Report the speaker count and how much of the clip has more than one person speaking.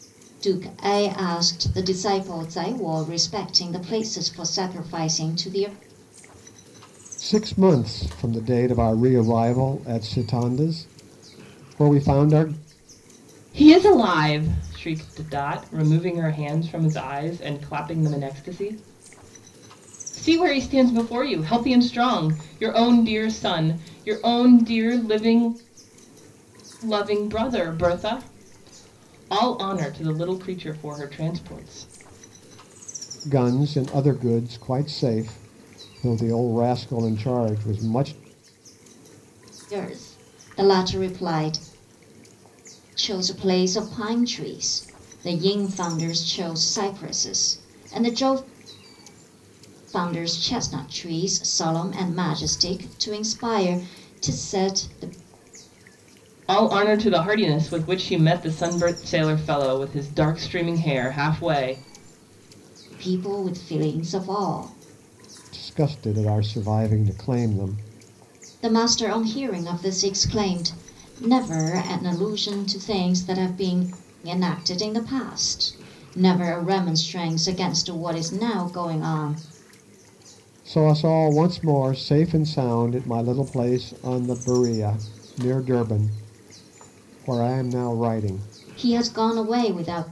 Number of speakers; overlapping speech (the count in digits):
3, no overlap